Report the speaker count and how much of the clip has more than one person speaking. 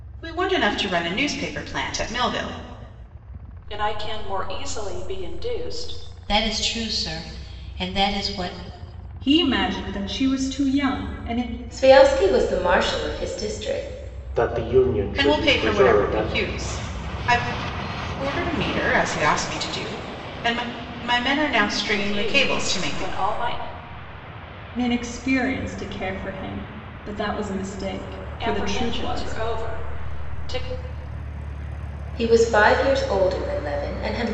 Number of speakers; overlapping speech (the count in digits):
6, about 10%